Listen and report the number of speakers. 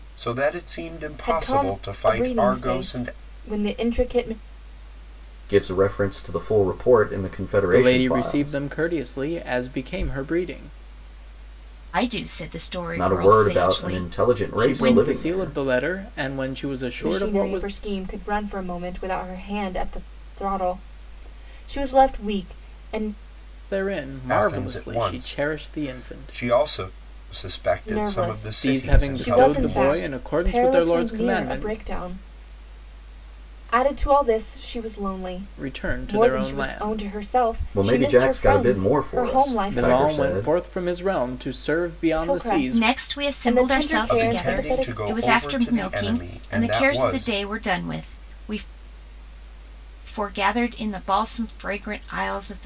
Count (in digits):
5